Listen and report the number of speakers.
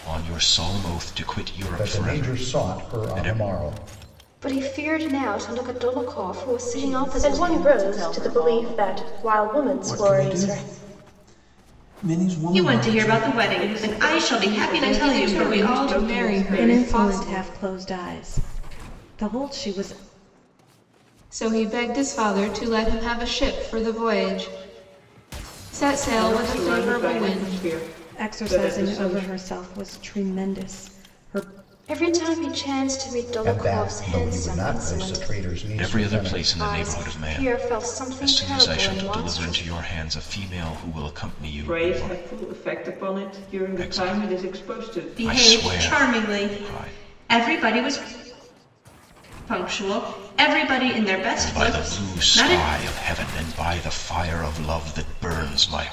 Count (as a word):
ten